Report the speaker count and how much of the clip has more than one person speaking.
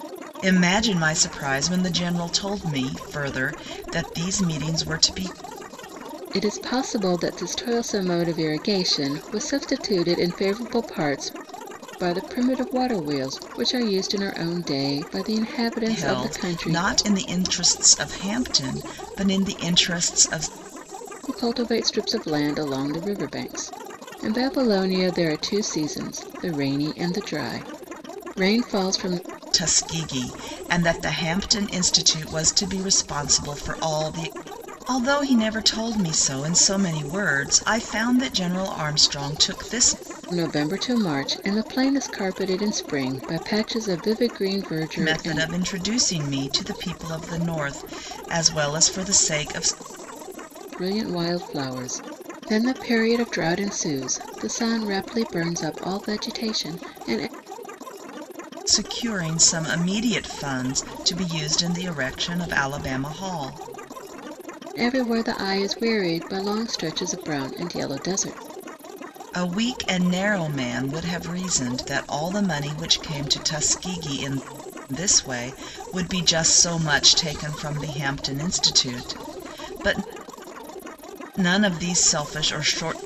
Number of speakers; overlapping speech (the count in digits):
2, about 2%